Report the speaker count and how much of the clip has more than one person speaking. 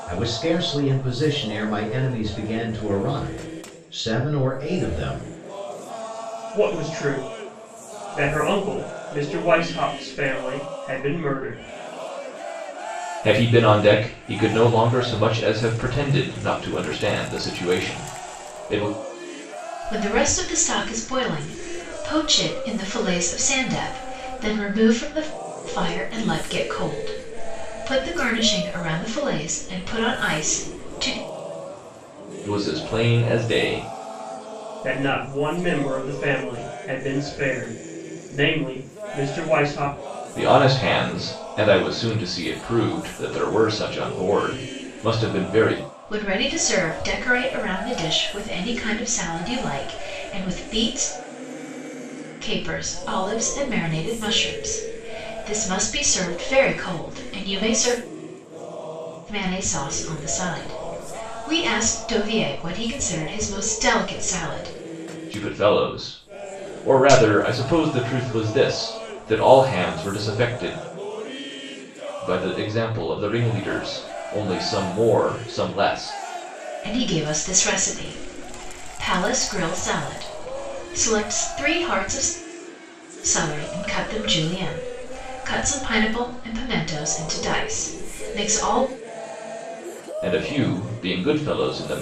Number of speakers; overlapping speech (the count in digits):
4, no overlap